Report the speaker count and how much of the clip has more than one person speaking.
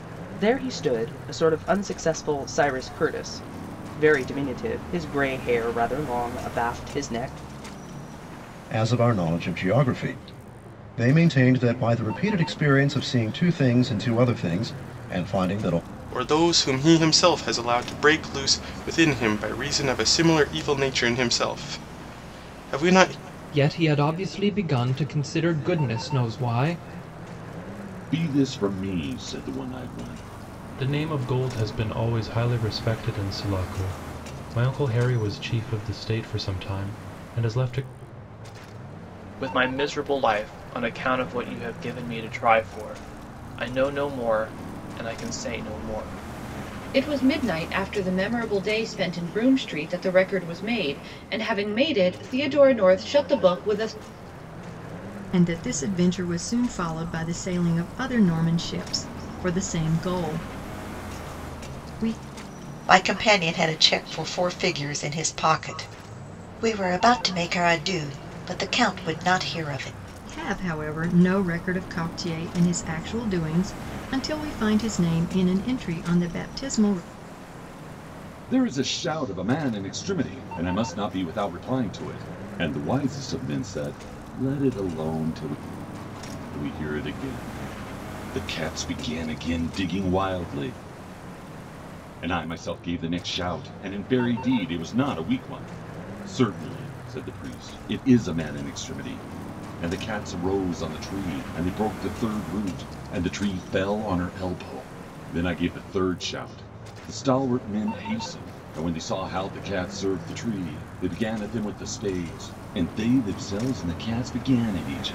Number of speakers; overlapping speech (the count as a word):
ten, no overlap